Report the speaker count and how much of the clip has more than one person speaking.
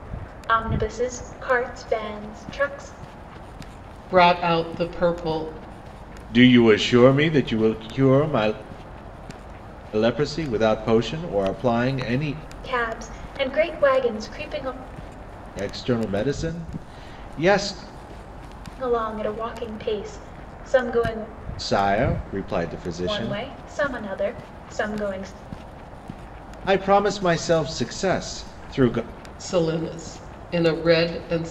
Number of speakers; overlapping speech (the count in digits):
3, about 1%